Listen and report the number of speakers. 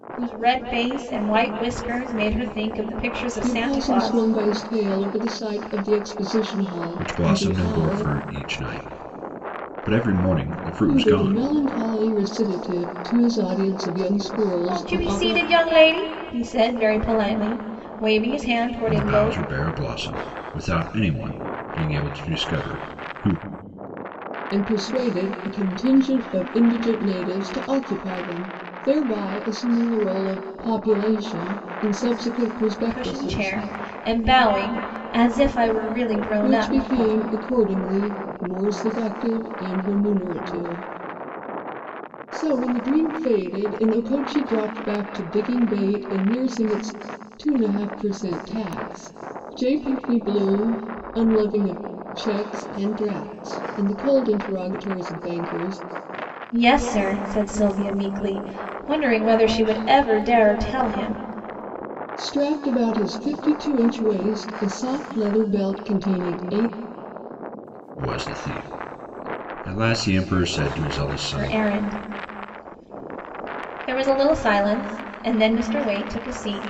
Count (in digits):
3